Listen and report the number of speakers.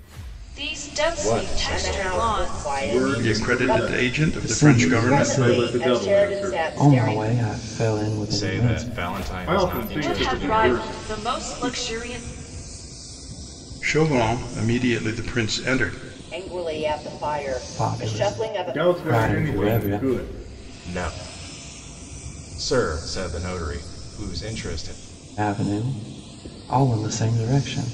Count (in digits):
6